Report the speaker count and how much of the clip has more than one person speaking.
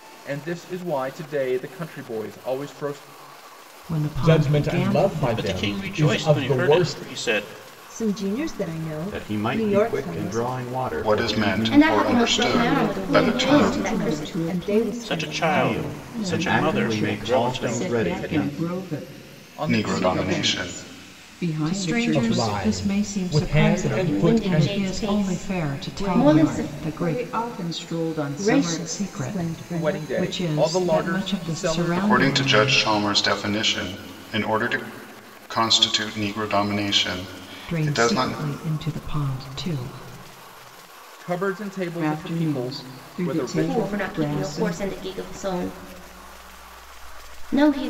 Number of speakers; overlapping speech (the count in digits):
9, about 57%